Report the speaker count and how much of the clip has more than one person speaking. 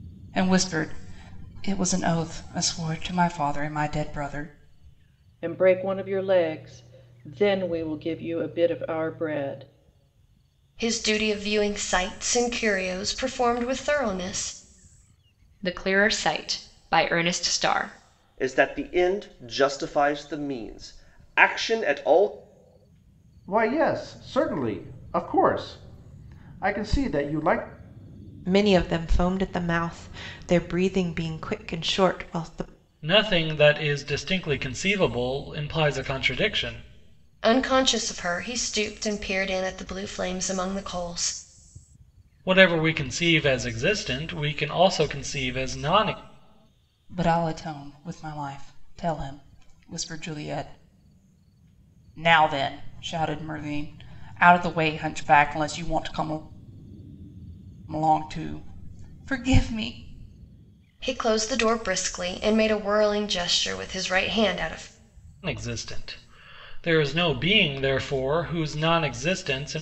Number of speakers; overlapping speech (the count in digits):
8, no overlap